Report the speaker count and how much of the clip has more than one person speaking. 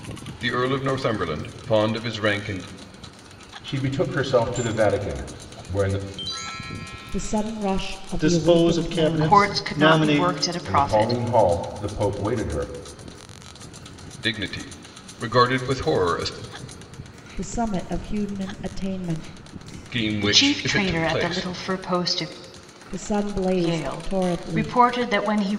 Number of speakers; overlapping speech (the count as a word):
five, about 21%